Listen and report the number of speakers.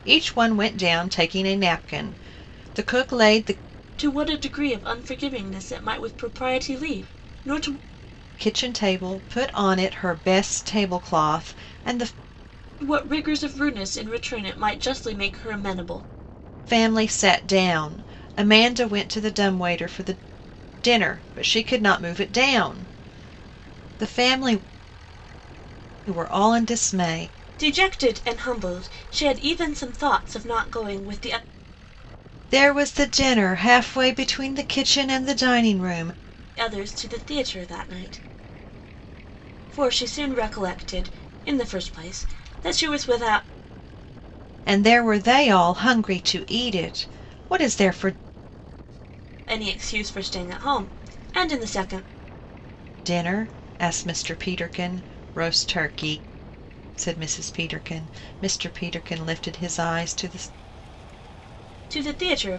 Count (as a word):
two